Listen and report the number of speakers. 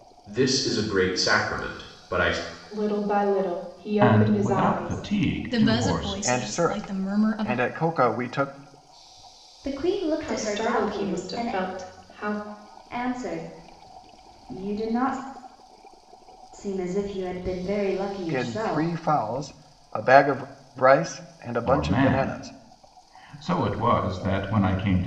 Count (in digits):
6